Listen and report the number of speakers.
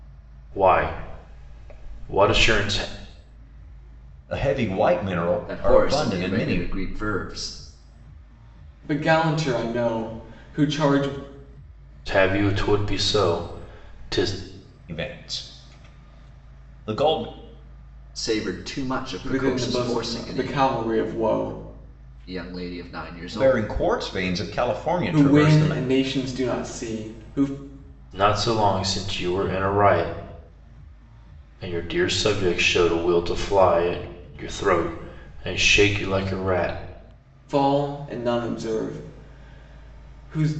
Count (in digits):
4